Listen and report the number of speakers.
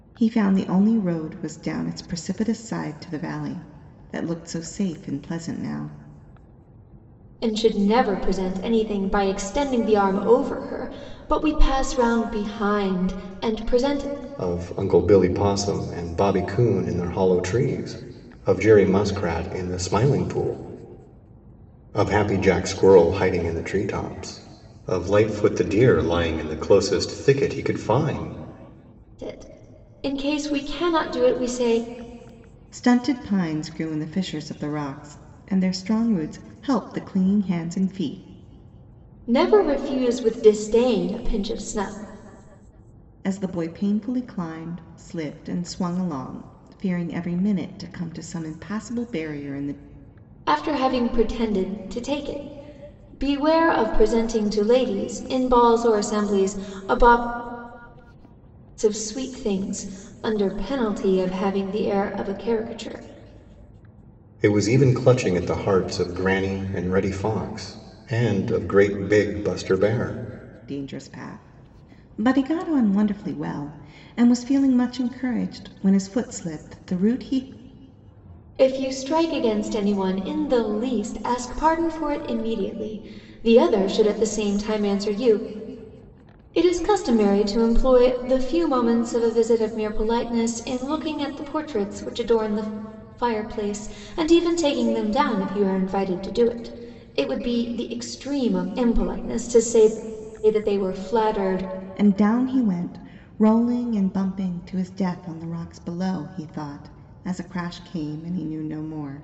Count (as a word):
three